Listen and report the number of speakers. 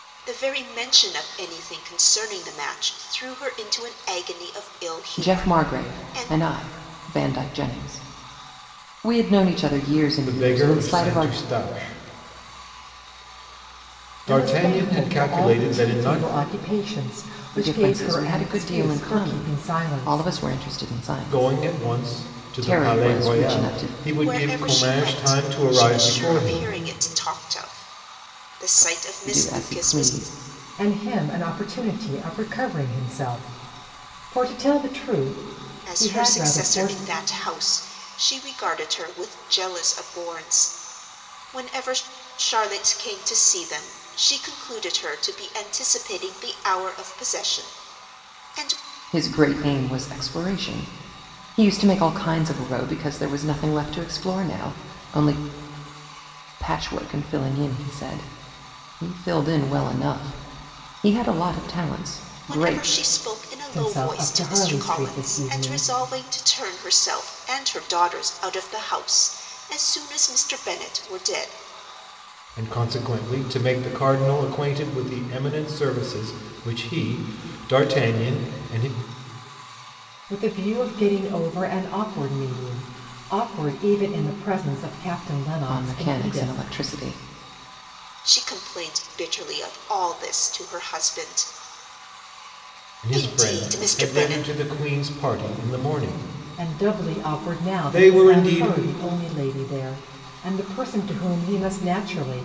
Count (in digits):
4